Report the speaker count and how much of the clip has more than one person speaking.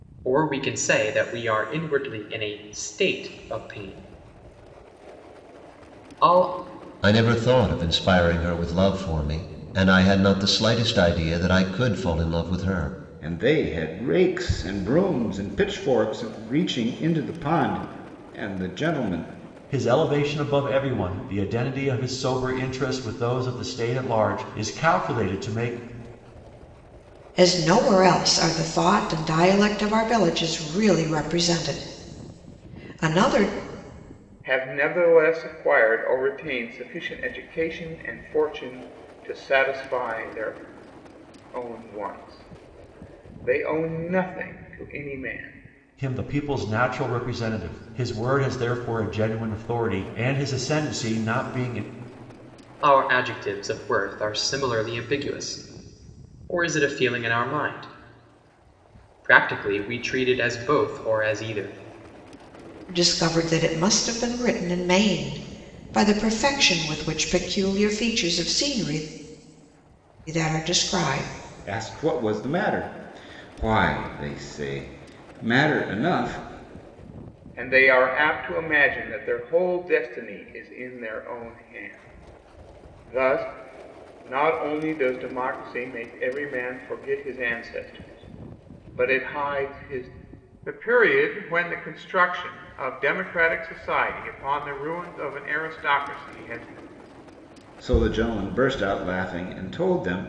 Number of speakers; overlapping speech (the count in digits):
6, no overlap